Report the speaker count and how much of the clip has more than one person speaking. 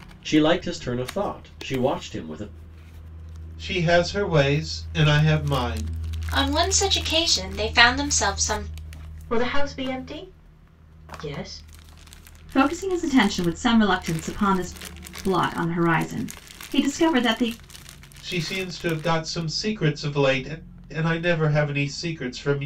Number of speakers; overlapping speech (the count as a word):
five, no overlap